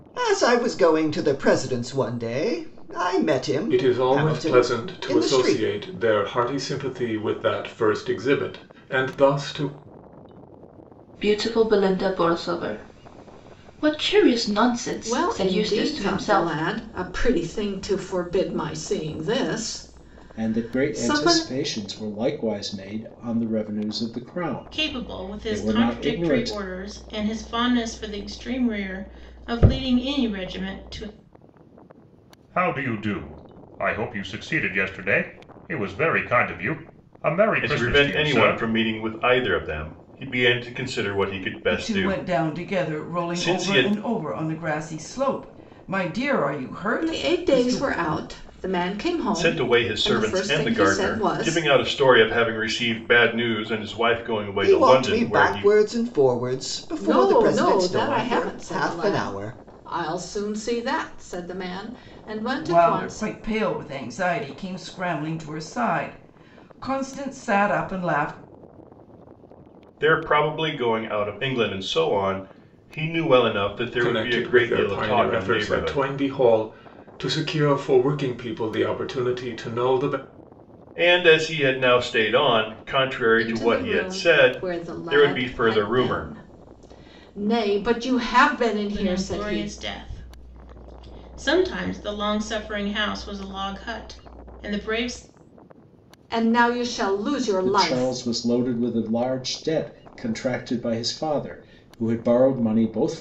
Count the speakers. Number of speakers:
9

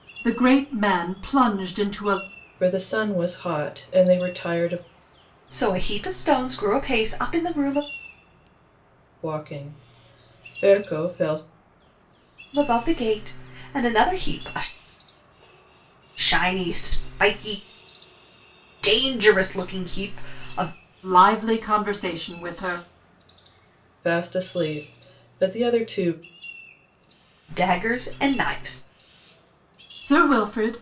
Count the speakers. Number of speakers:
3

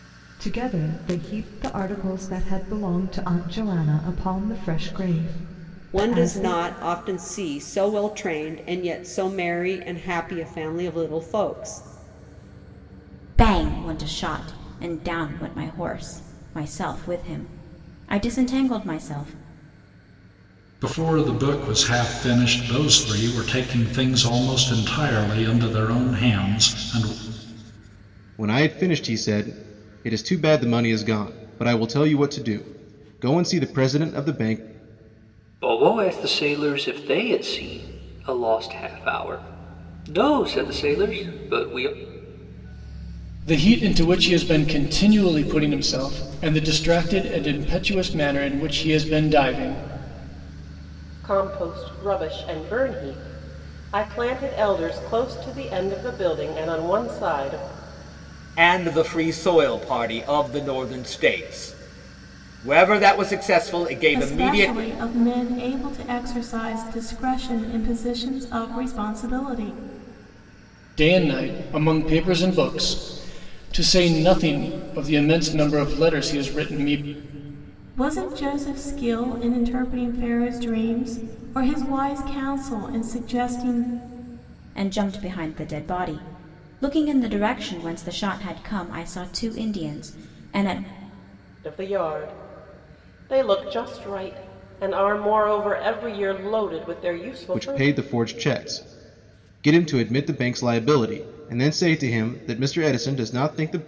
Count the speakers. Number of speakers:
10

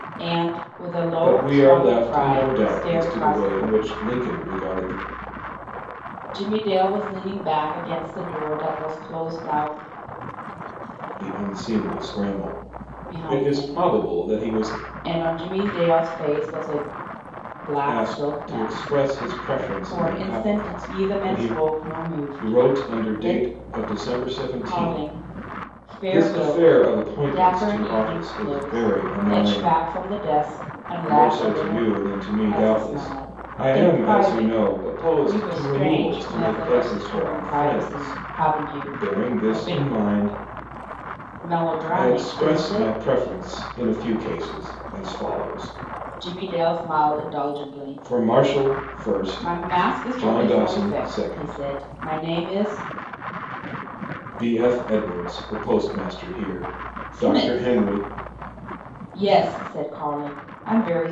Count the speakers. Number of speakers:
2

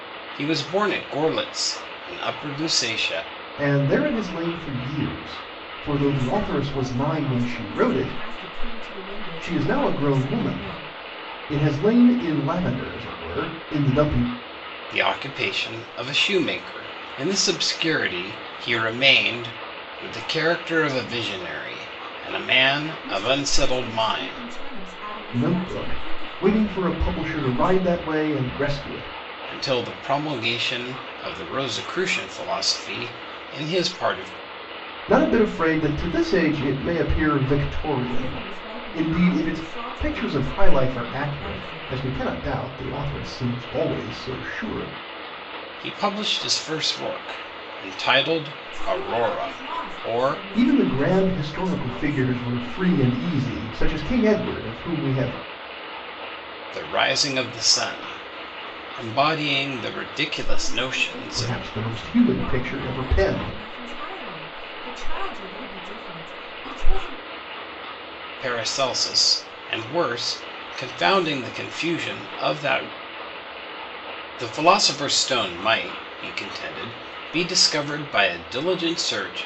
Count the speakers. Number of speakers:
3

